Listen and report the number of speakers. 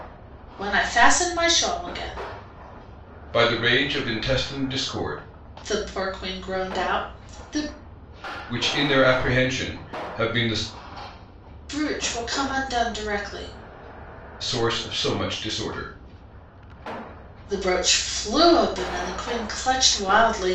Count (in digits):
2